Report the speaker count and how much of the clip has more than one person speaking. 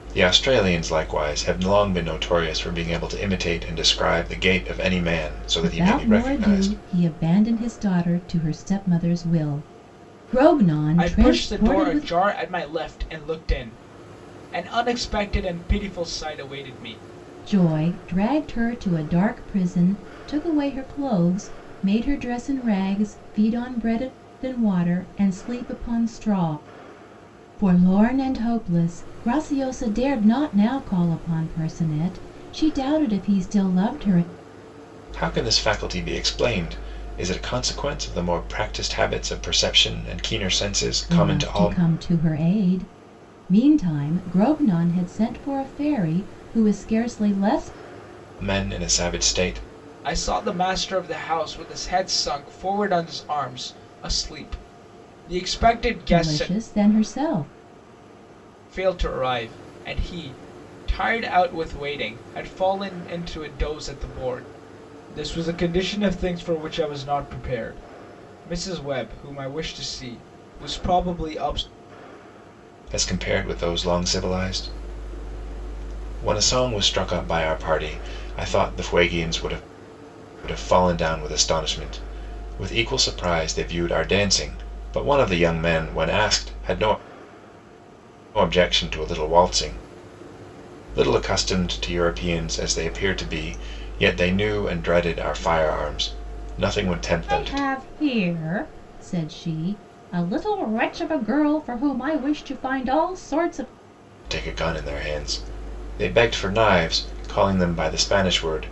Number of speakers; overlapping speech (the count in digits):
3, about 4%